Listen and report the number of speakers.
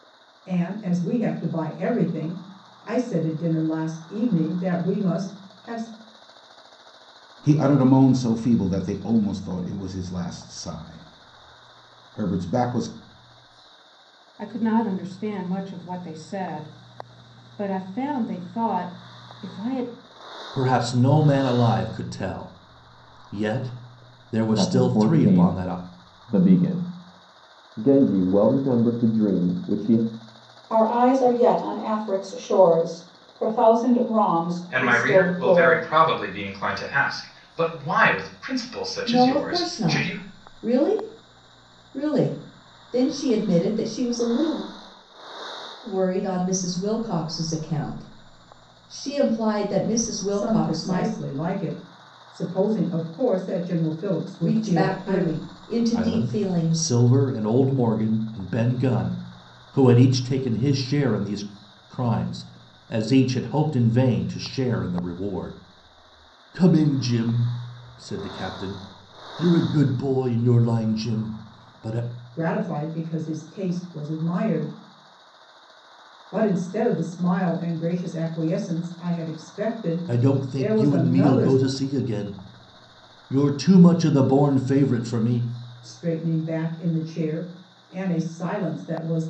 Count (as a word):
eight